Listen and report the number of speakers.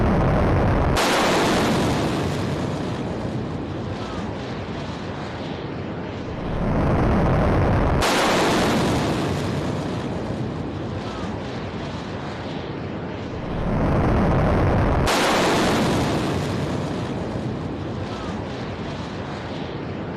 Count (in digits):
0